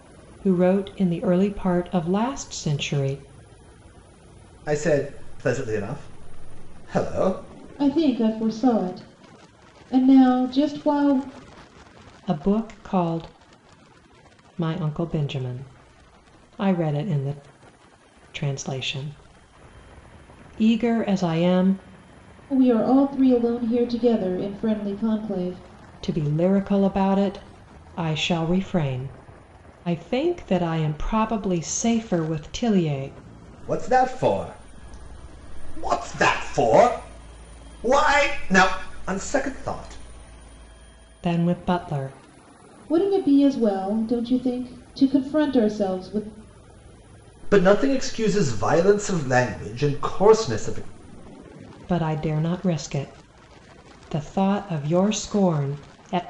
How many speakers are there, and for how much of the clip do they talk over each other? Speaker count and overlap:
3, no overlap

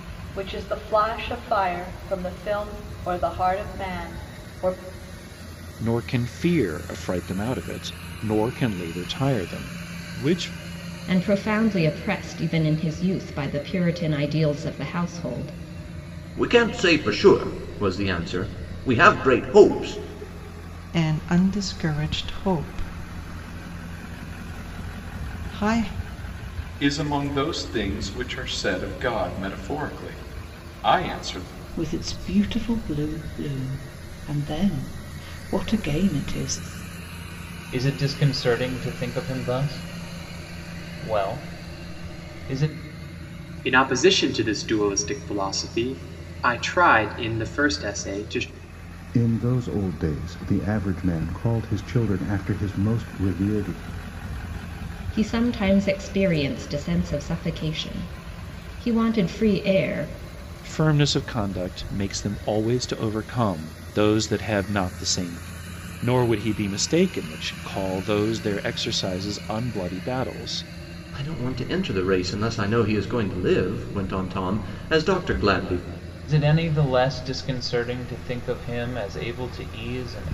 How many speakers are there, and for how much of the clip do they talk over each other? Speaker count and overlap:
10, no overlap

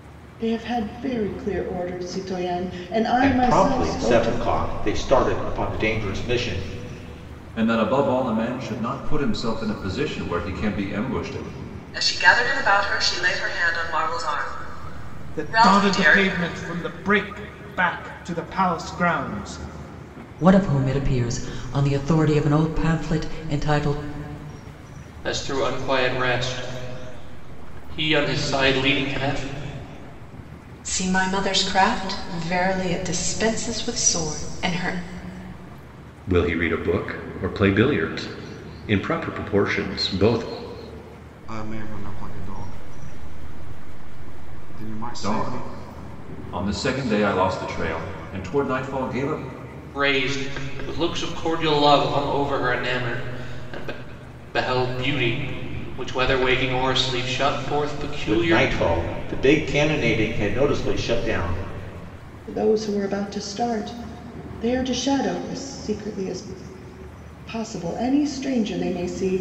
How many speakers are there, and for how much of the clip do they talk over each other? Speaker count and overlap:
10, about 5%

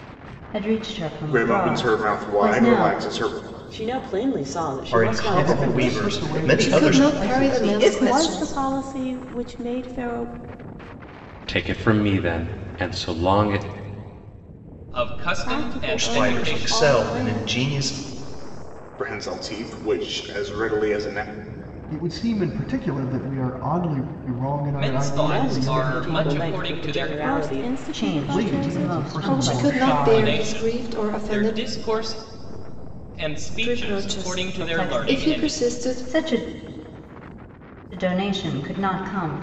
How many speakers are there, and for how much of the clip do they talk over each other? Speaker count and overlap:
10, about 43%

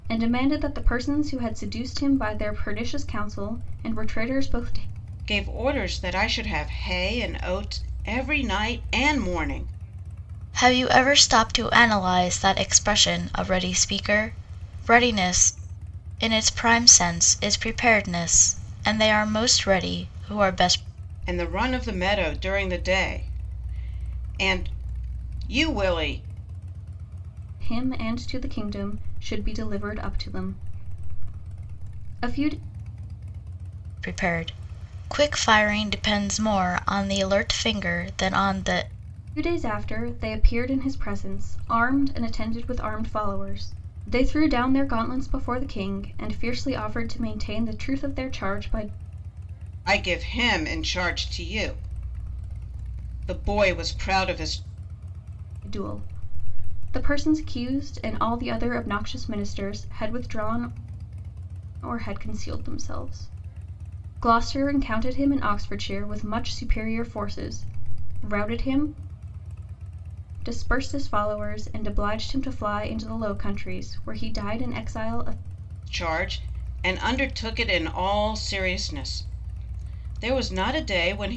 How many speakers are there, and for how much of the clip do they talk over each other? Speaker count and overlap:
3, no overlap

